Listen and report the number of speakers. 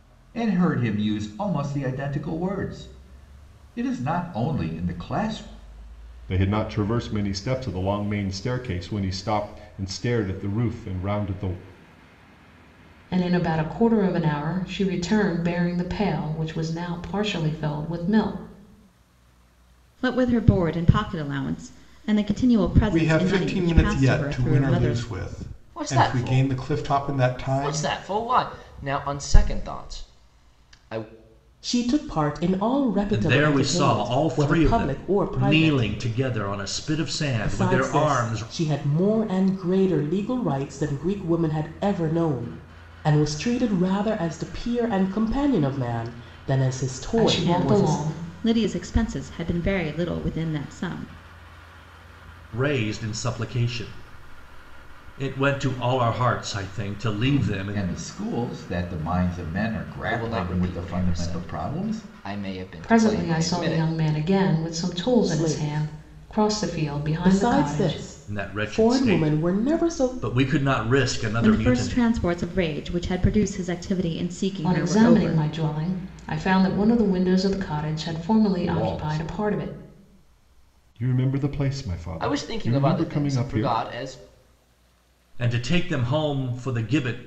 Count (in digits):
8